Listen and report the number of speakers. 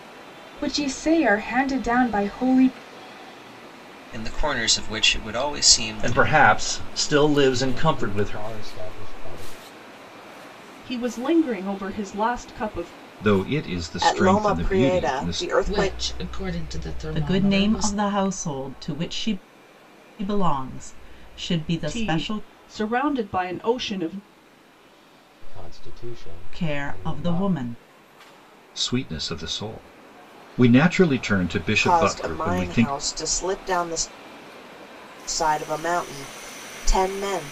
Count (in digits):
9